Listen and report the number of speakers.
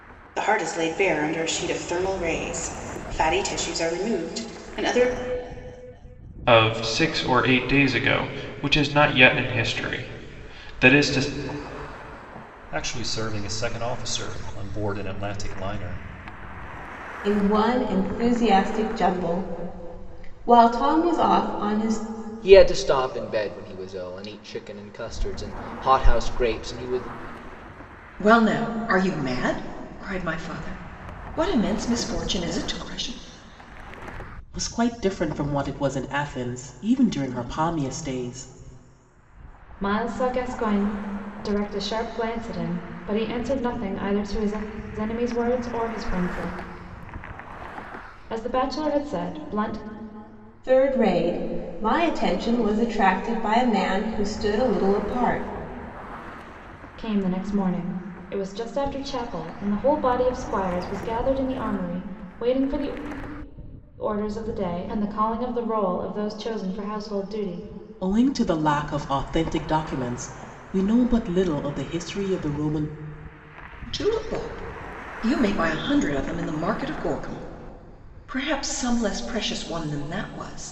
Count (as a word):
eight